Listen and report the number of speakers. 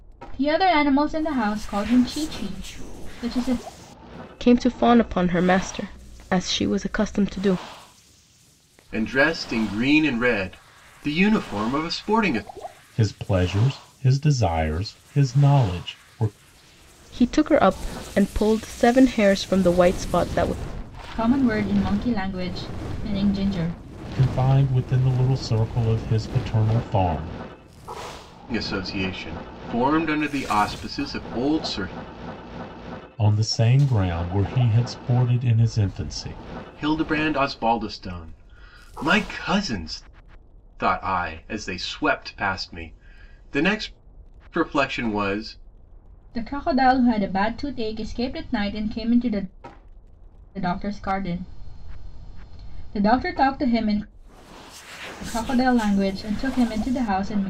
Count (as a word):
four